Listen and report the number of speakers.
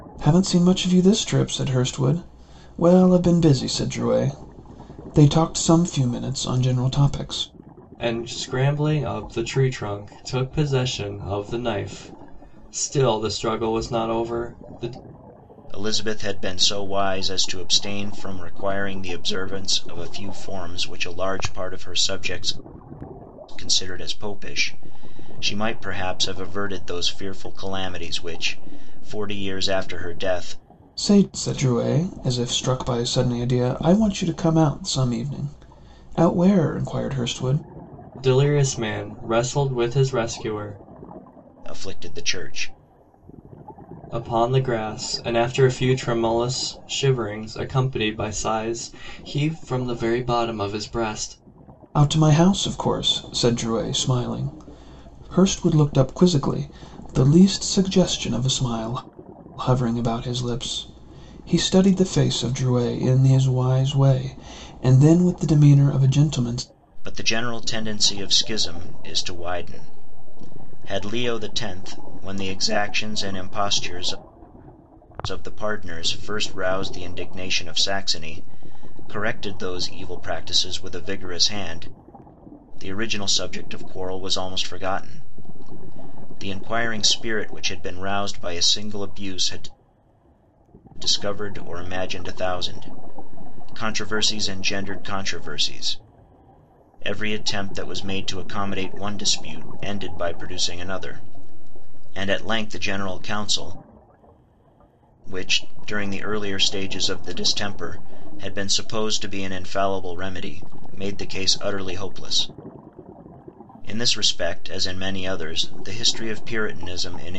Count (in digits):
3